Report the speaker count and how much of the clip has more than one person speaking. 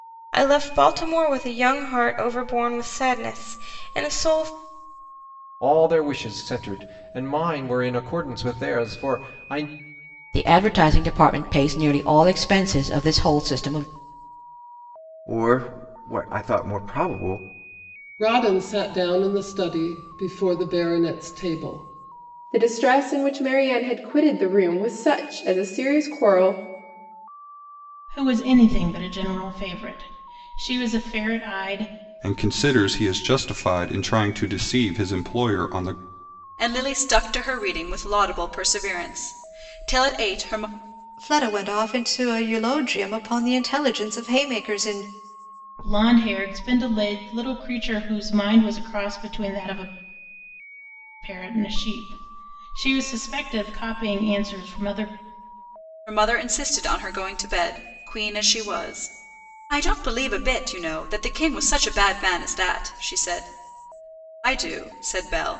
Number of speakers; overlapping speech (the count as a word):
ten, no overlap